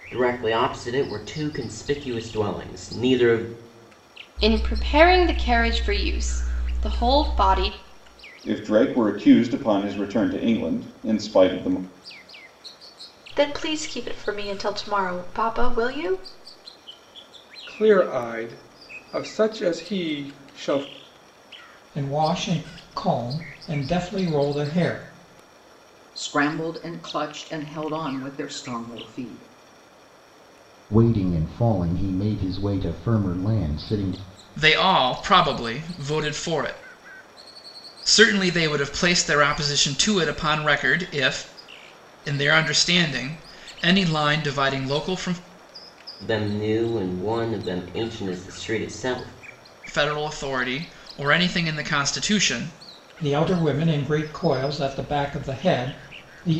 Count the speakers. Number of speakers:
9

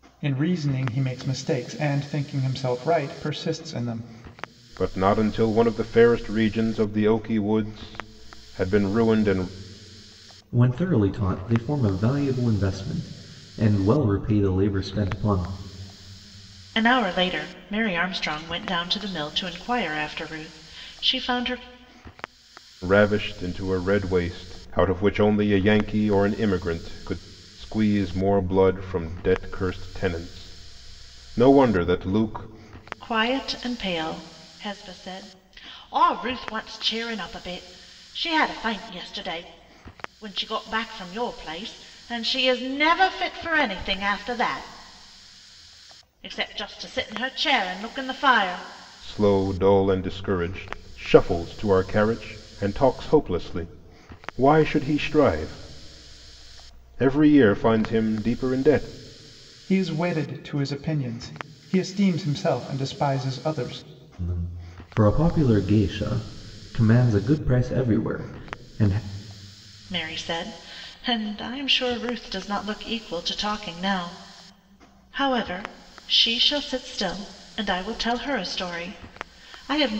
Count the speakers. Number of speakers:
4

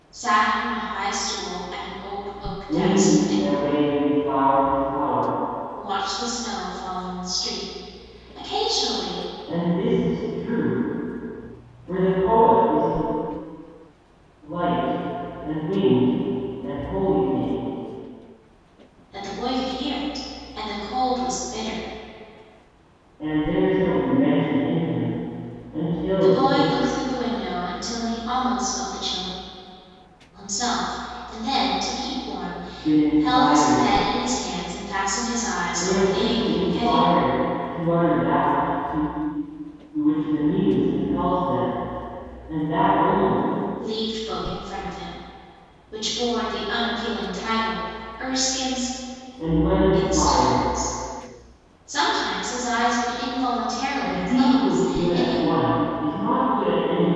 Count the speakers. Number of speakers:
2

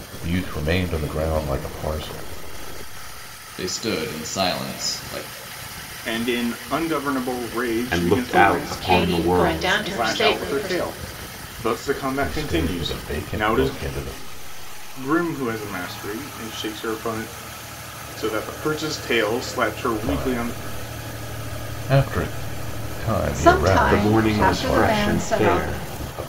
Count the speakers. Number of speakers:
6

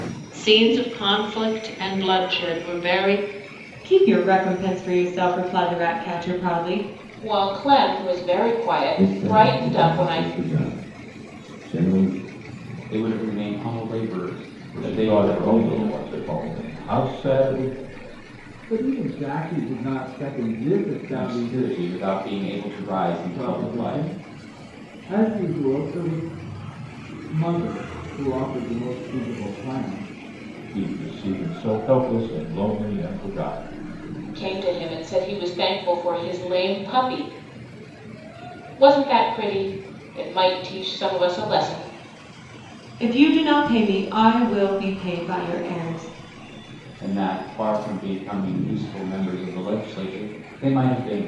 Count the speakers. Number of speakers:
7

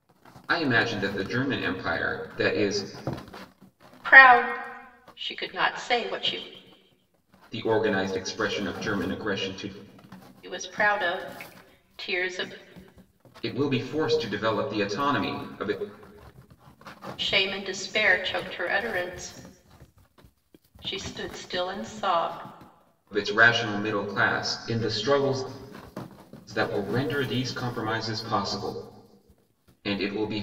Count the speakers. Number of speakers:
2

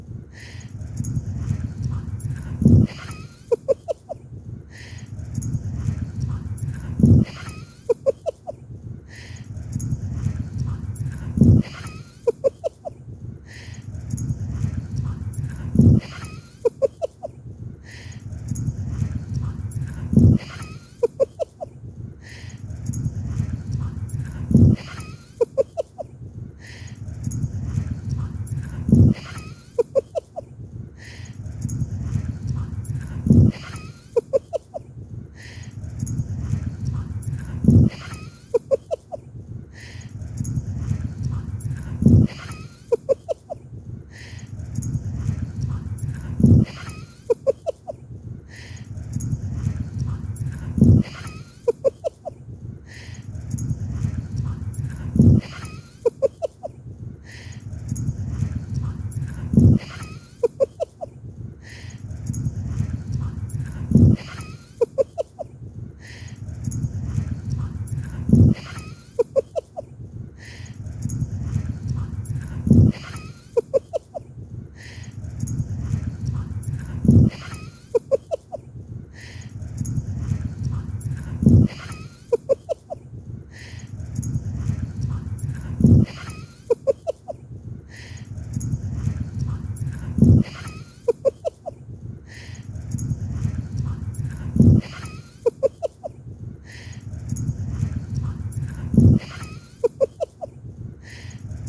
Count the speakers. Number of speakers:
0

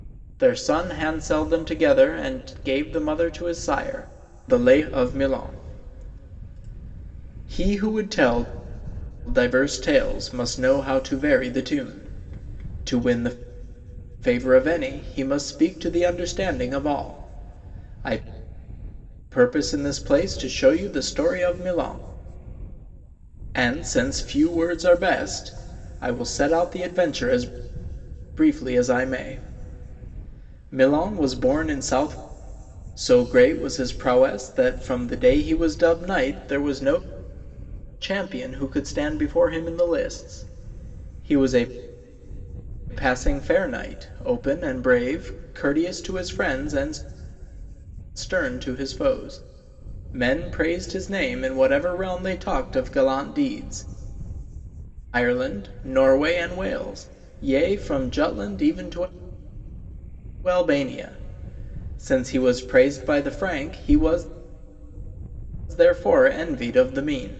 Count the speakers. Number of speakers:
1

